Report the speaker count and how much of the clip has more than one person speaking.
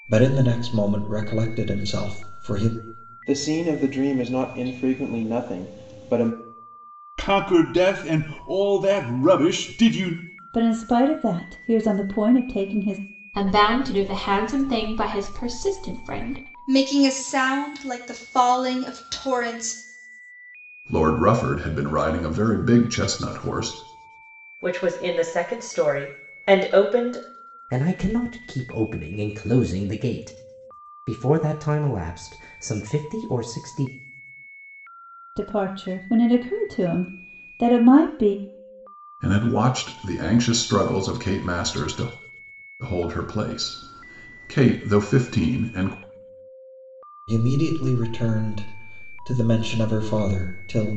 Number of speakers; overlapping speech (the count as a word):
nine, no overlap